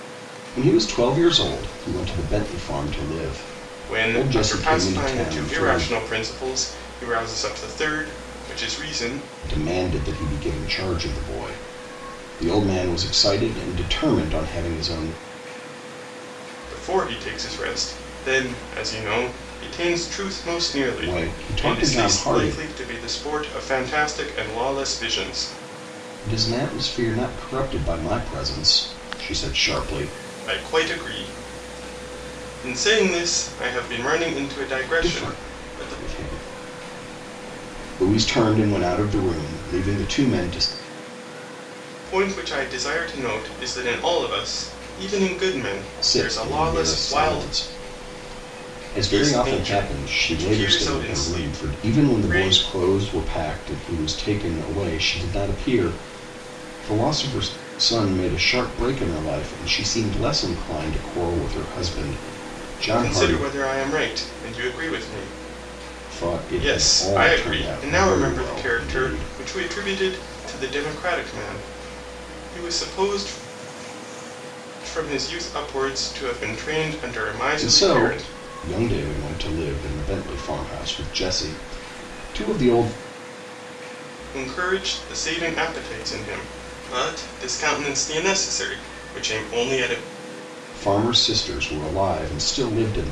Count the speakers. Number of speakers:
two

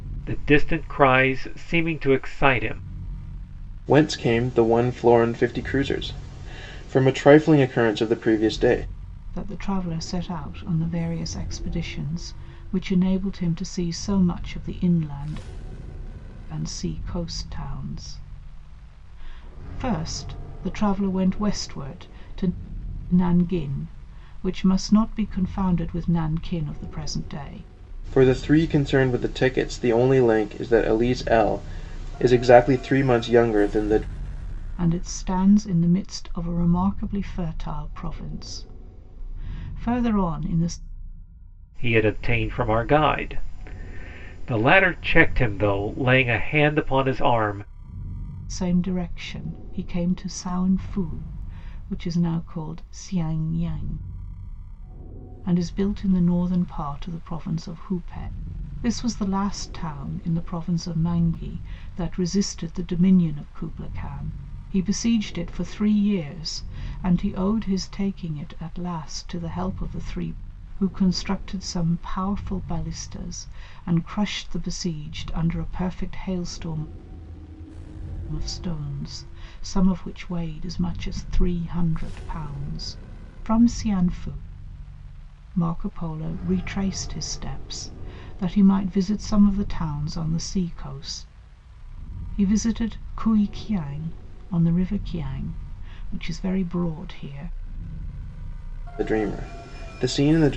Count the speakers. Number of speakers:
three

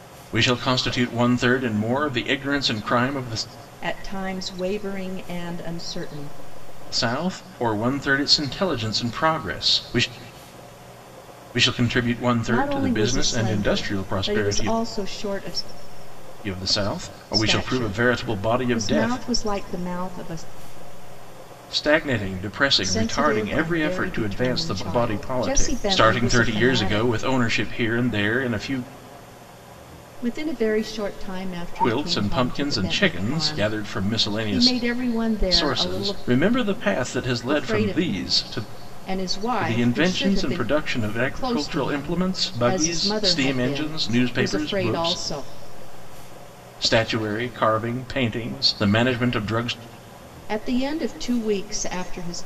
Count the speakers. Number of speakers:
two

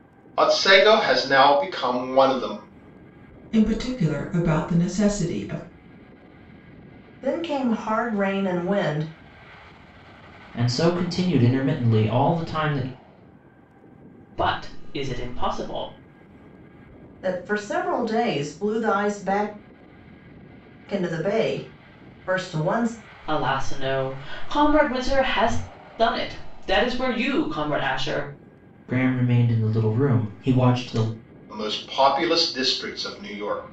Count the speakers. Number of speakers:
five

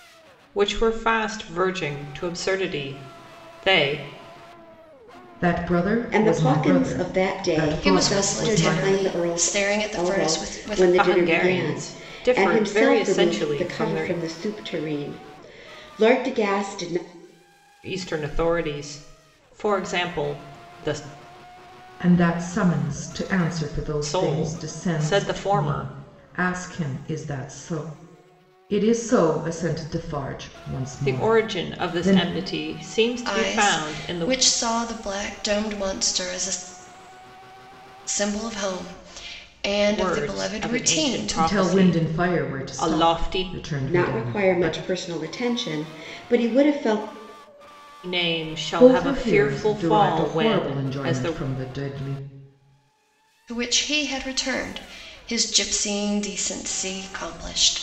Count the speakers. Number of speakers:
four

